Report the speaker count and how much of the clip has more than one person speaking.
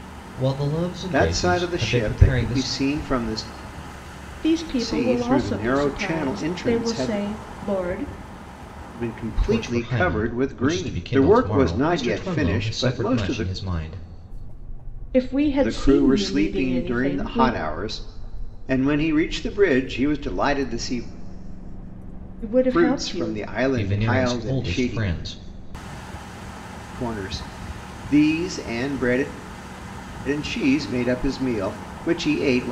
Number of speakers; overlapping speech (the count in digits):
3, about 37%